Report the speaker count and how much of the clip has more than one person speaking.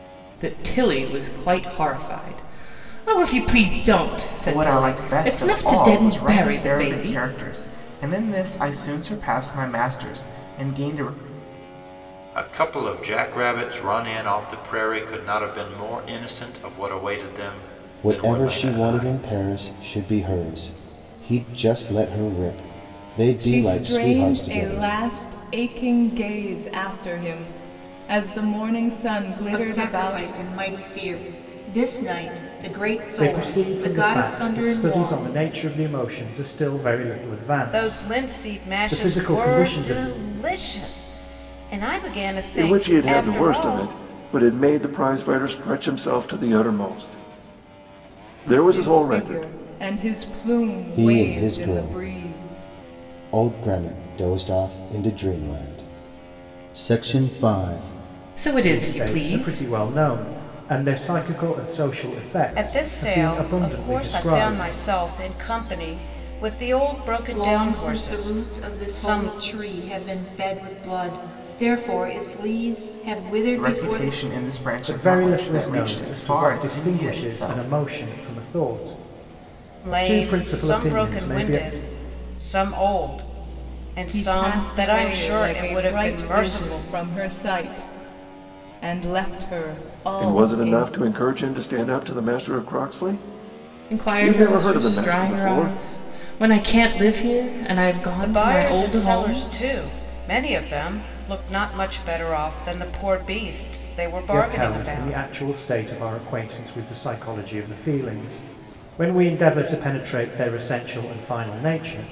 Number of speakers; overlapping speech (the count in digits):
9, about 30%